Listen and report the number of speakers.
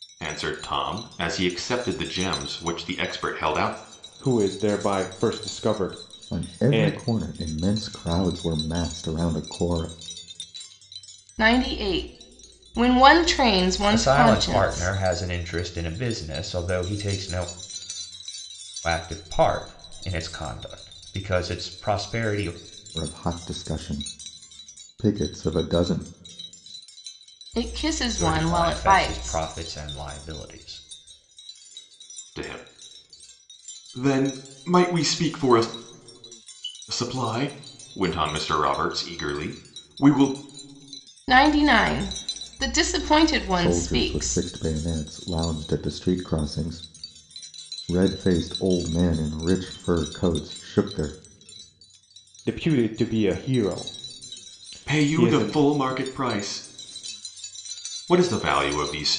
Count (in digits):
5